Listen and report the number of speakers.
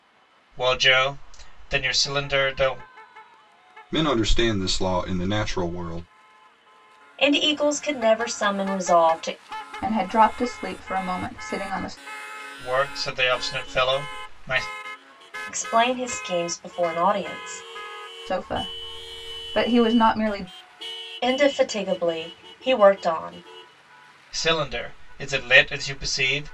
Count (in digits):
4